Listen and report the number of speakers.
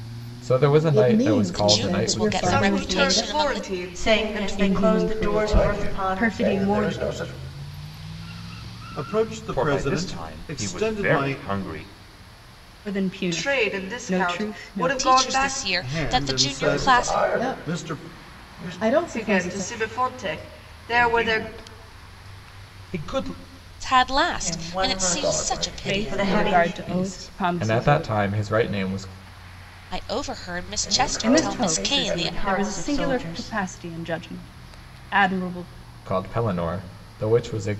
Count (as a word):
nine